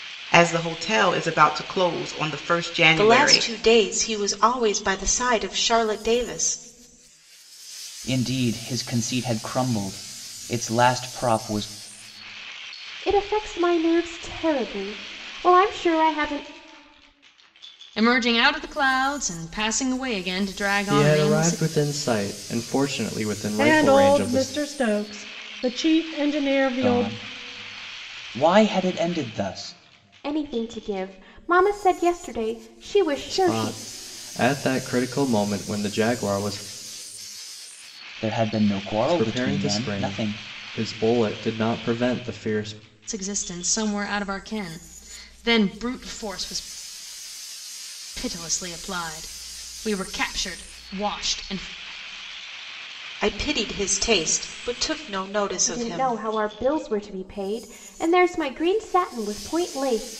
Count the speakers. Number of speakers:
7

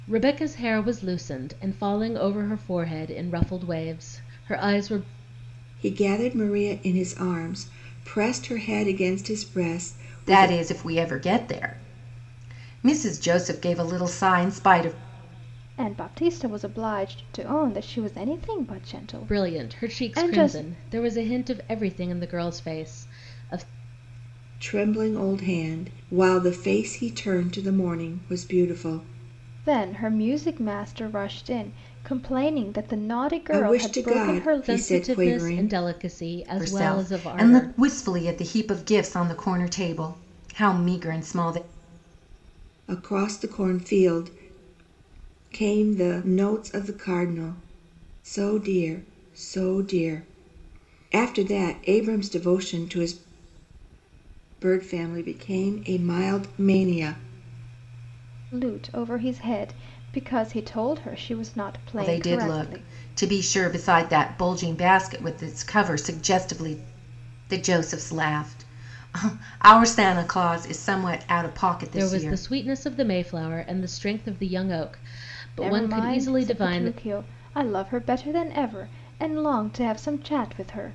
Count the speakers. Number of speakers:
4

